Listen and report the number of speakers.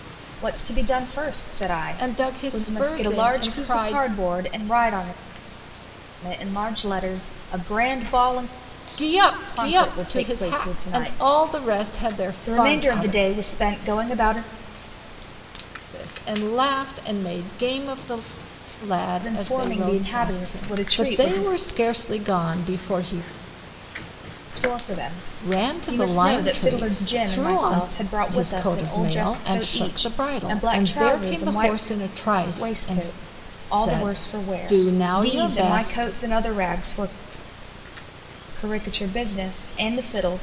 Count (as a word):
two